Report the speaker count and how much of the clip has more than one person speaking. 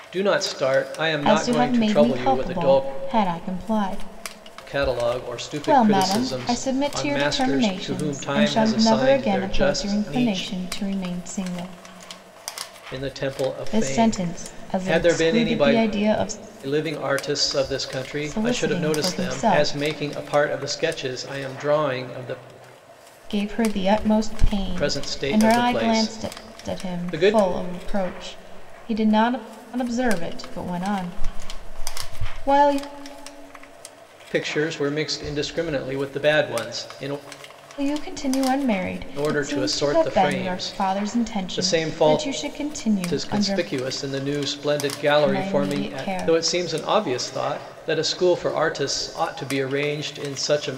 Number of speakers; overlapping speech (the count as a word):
two, about 35%